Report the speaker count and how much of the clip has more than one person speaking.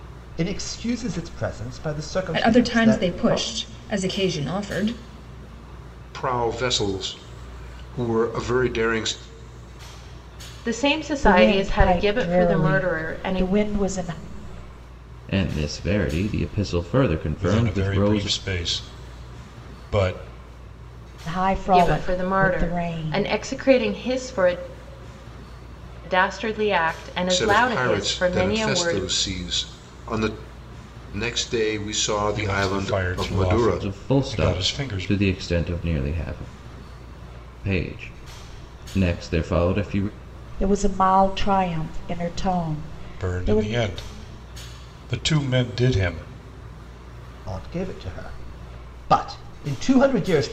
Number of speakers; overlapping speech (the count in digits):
7, about 23%